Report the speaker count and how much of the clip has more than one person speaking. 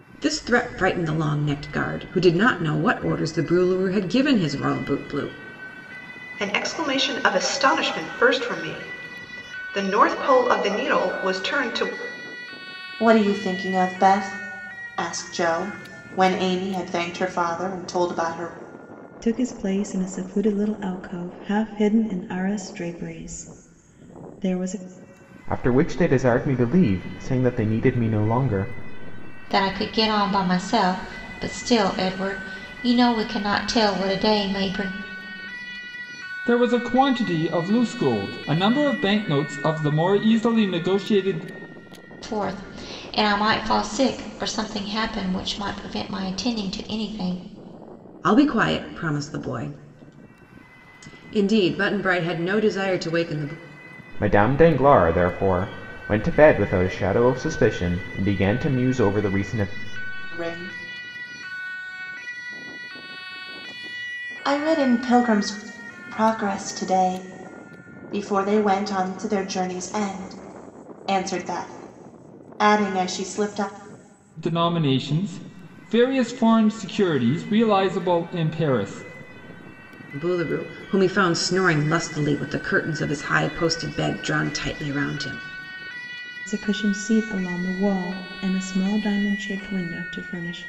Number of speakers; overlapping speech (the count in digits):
7, no overlap